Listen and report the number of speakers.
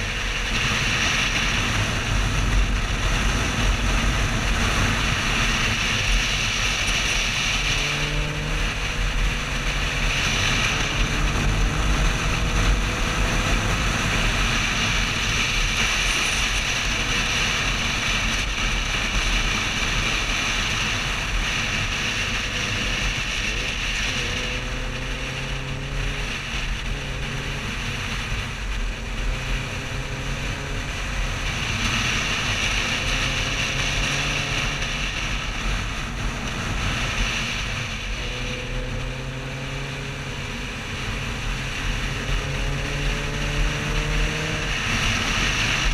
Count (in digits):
0